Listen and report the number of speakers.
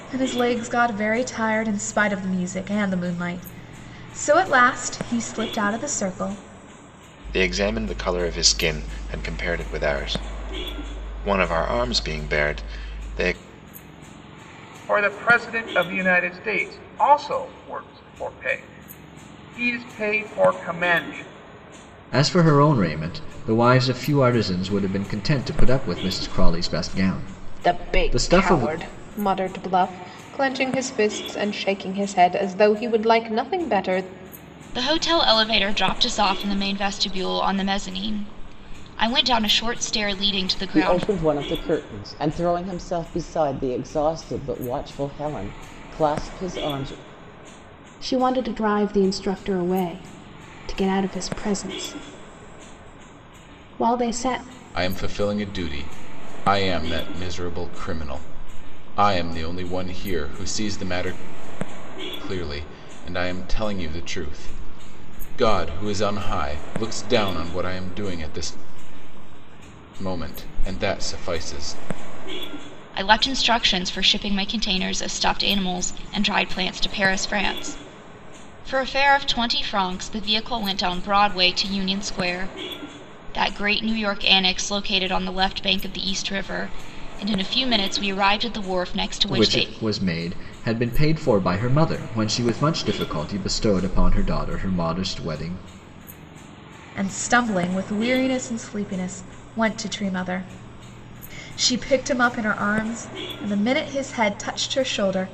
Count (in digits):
9